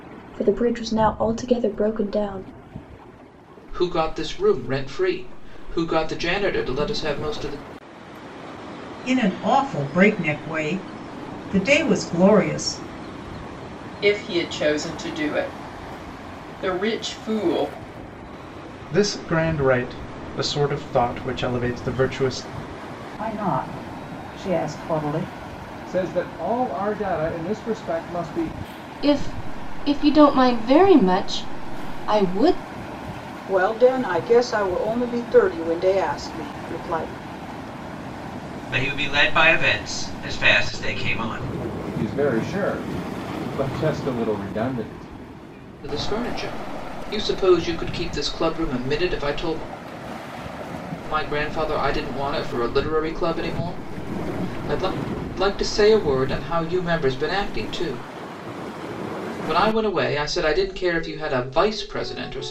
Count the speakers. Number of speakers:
10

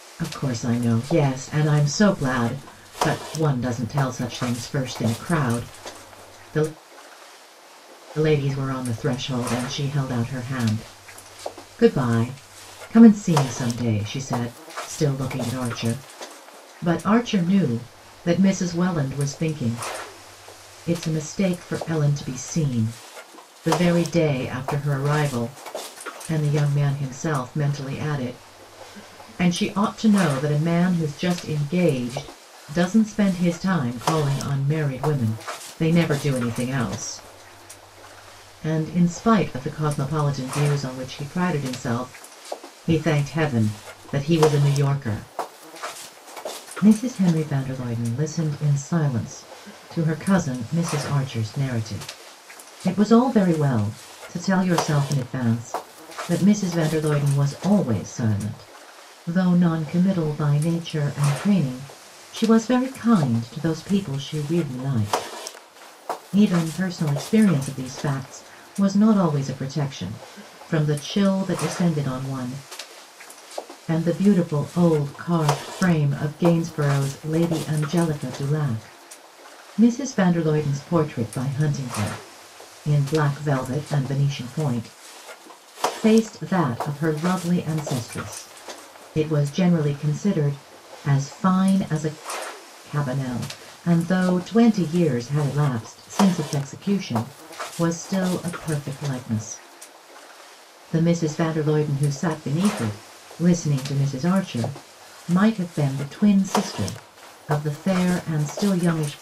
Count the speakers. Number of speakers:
1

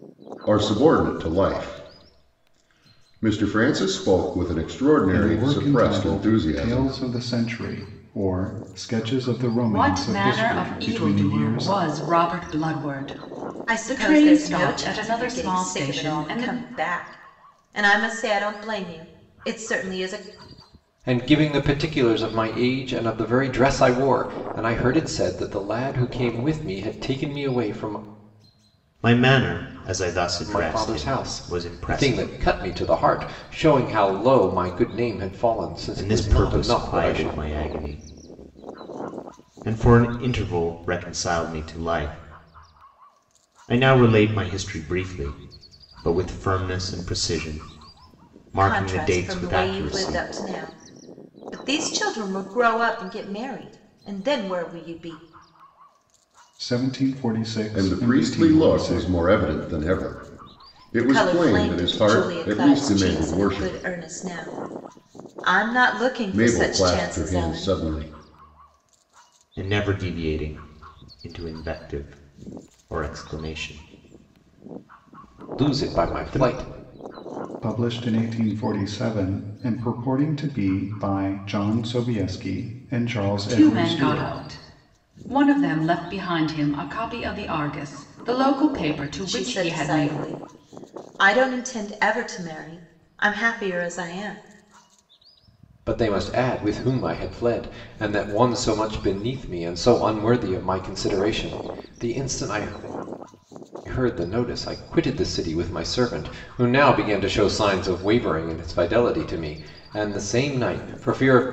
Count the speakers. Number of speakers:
6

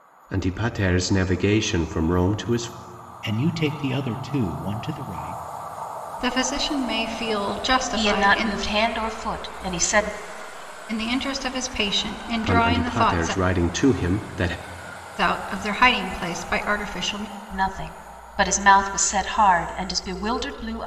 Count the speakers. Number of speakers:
4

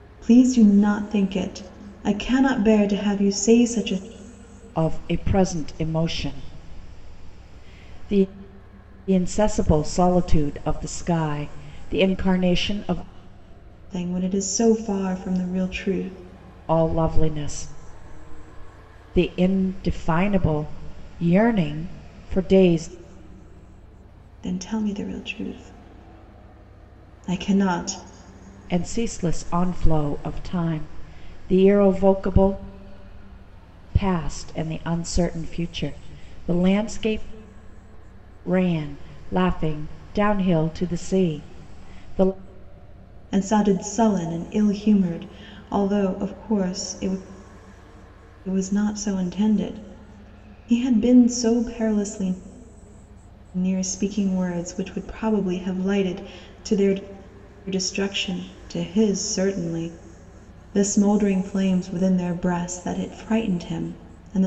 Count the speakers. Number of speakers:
2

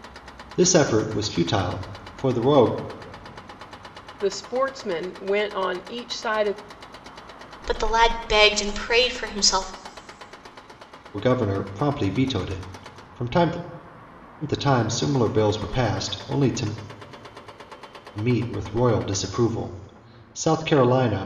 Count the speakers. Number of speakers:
3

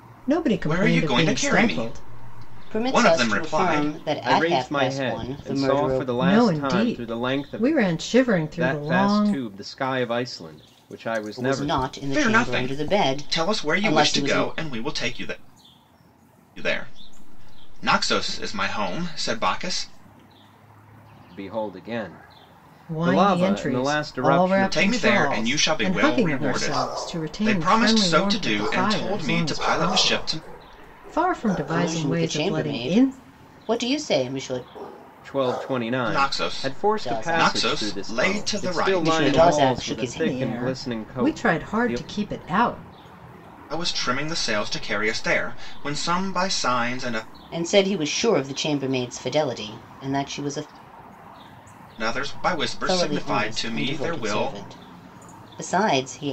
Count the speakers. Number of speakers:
4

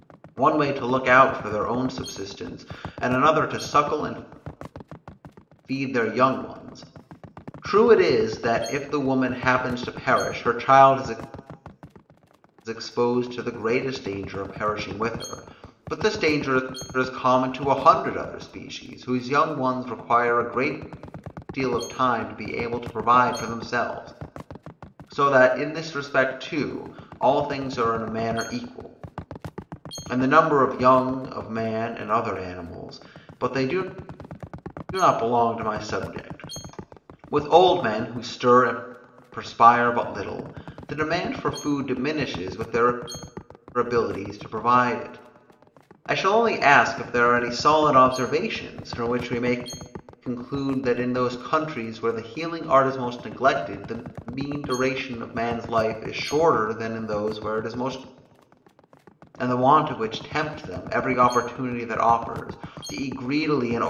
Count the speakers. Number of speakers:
1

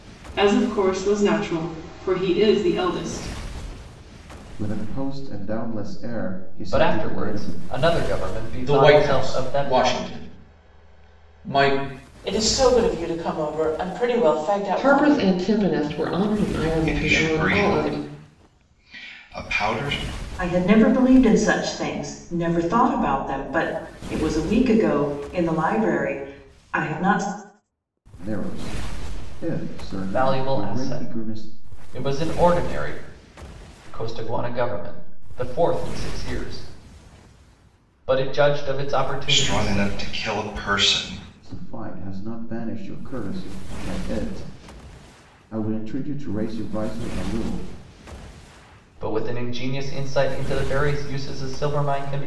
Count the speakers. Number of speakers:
8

